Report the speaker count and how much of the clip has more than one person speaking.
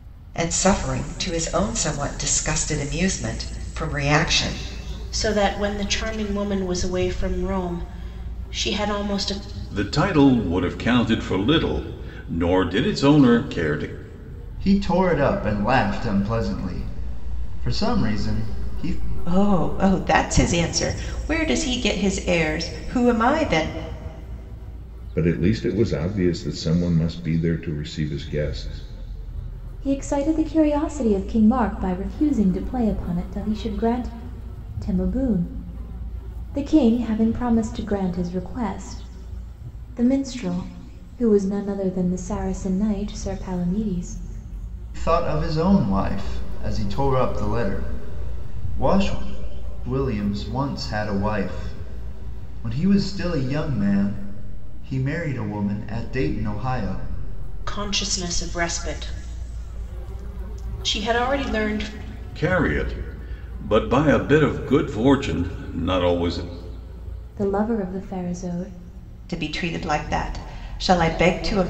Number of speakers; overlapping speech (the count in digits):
7, no overlap